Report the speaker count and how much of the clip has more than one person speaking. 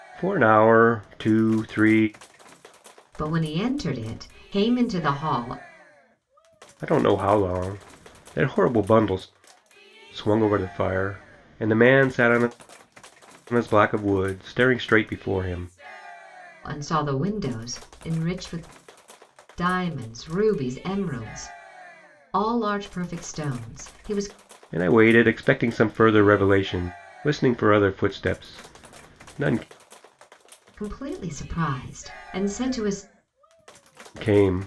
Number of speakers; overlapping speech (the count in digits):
2, no overlap